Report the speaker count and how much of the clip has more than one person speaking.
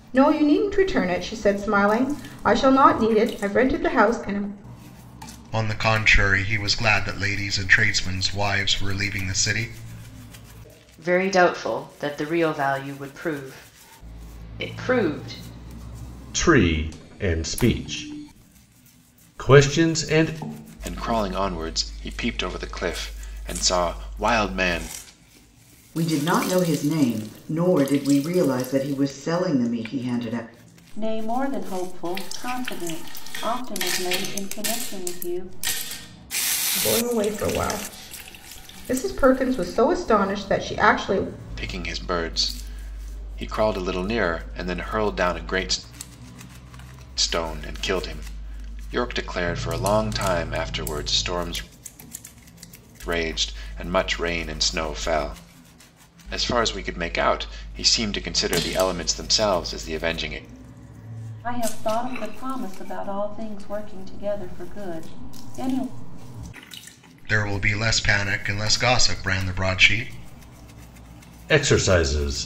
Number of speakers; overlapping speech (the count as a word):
seven, no overlap